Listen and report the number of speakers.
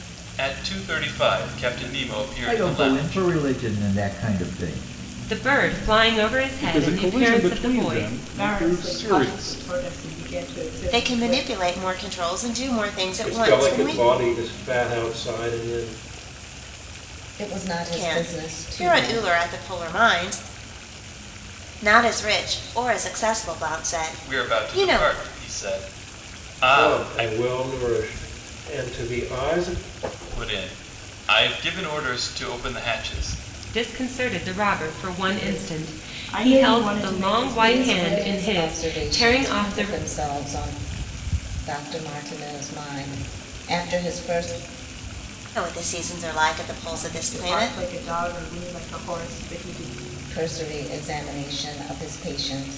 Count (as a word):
eight